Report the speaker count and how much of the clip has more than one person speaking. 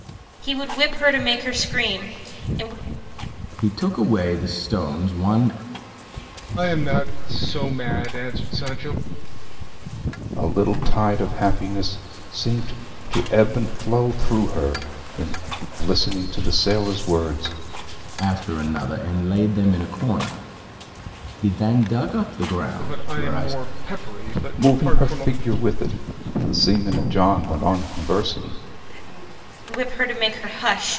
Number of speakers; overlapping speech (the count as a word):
four, about 5%